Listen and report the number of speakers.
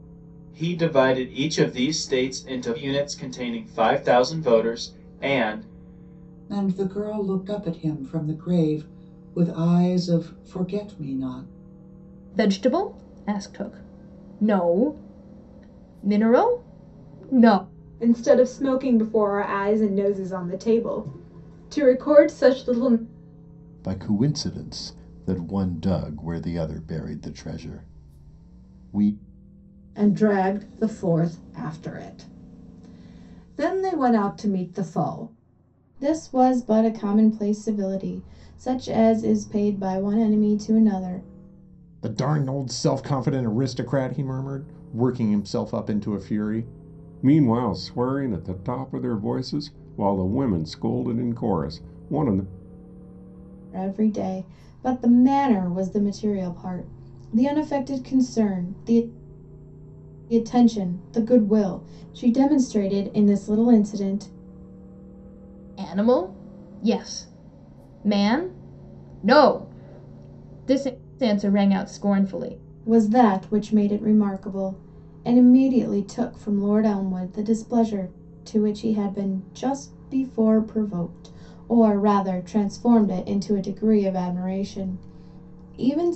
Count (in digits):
9